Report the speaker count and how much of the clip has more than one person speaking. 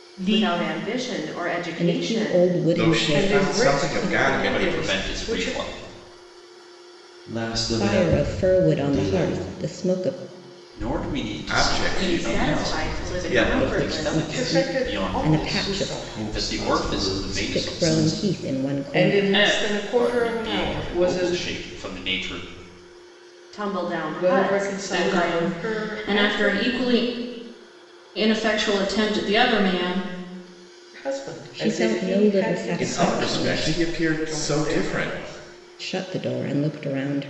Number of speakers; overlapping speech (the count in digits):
7, about 56%